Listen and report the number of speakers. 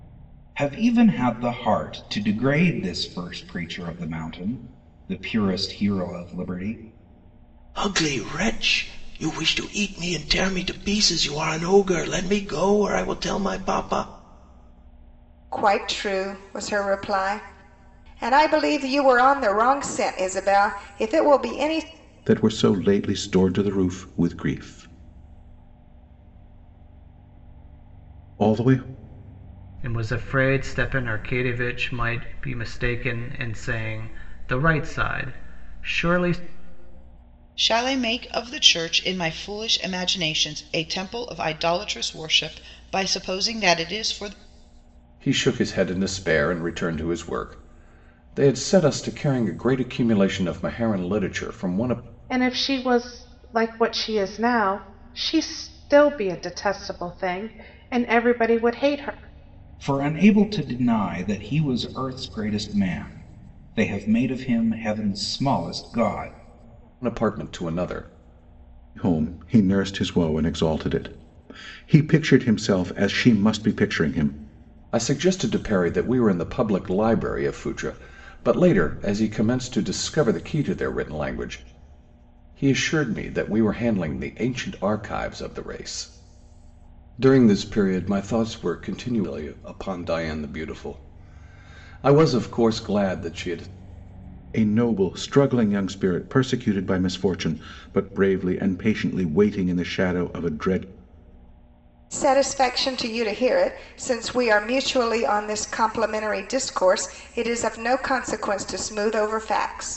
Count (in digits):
8